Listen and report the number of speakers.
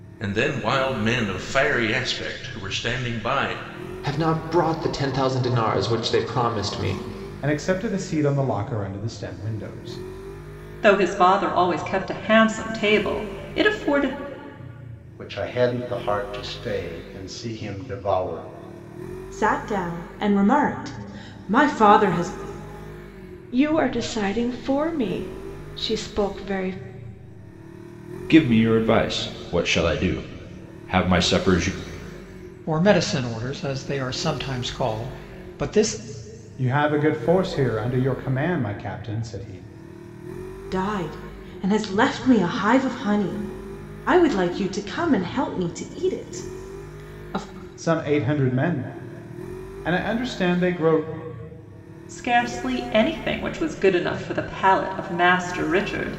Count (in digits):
9